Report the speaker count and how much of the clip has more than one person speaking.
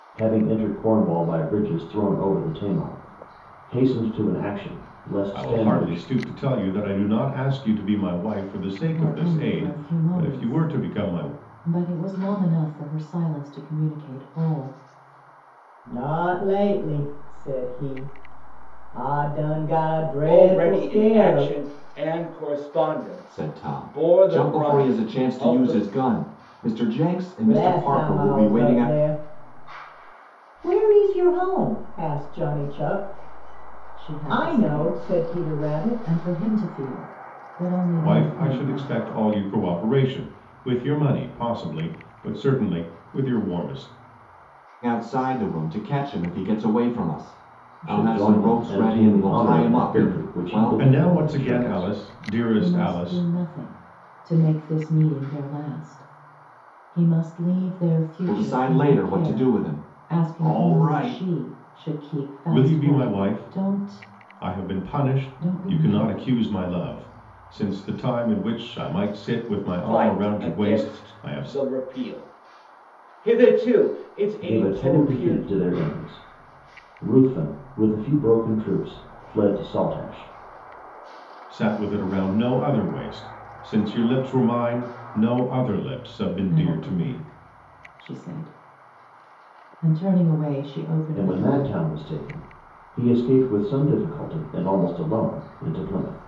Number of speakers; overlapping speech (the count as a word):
six, about 28%